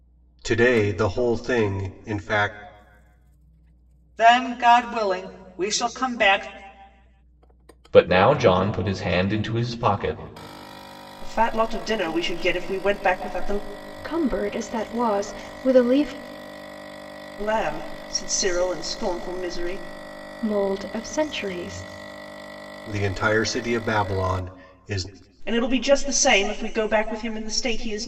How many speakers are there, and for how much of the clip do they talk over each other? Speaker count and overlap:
five, no overlap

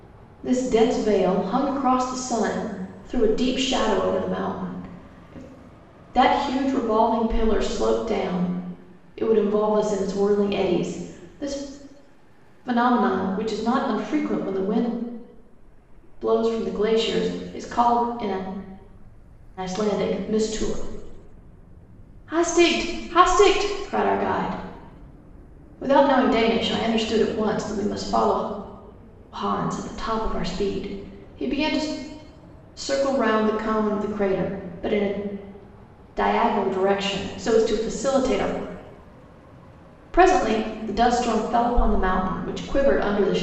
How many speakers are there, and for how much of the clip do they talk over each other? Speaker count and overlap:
one, no overlap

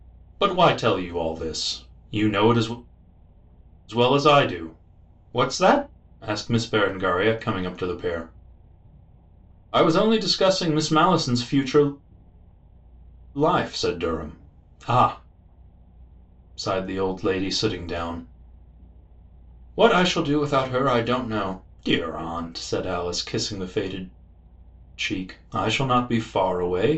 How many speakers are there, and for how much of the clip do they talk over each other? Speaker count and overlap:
one, no overlap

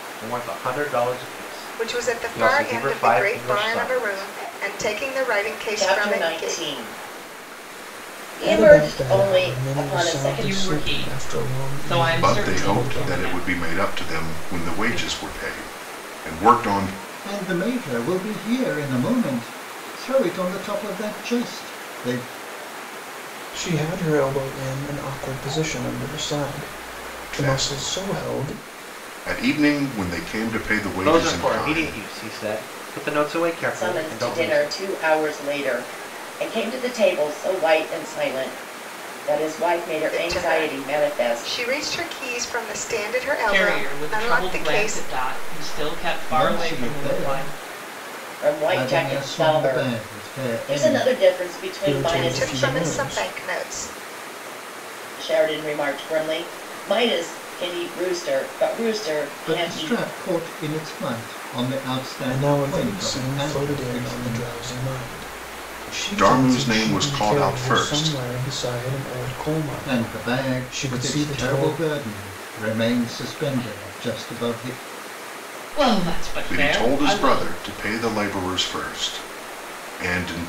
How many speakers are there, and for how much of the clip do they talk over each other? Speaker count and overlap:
seven, about 38%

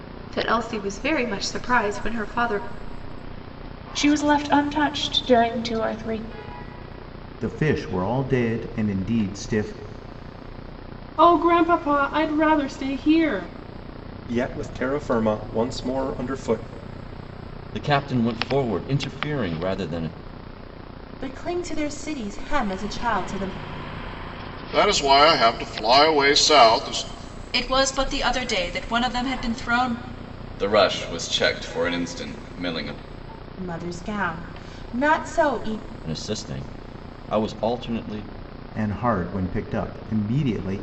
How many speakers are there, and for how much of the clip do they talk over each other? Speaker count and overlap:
ten, no overlap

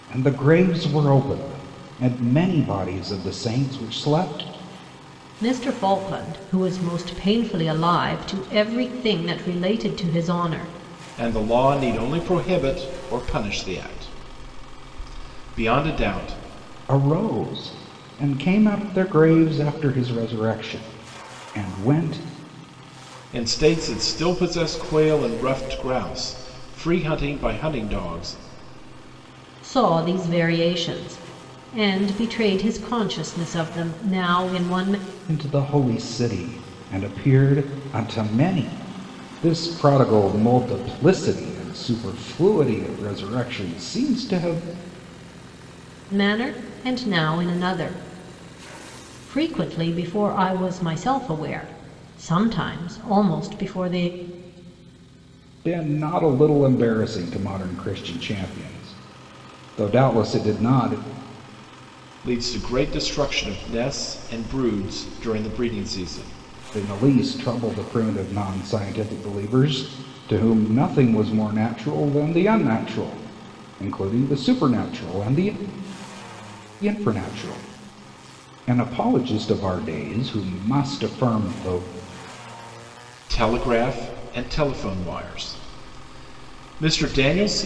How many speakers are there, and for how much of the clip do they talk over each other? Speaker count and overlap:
three, no overlap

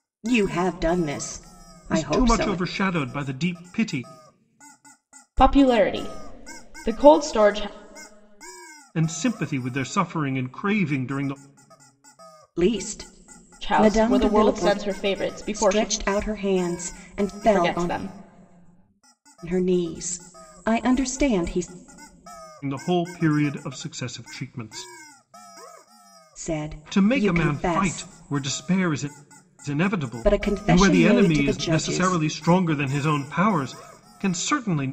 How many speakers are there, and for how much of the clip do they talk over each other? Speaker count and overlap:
three, about 18%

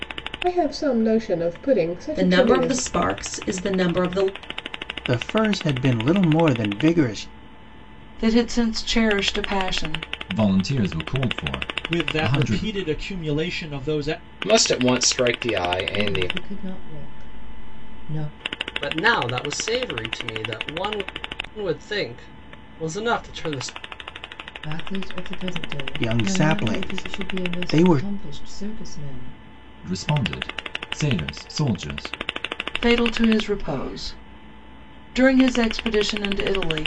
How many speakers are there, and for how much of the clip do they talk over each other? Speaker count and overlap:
nine, about 11%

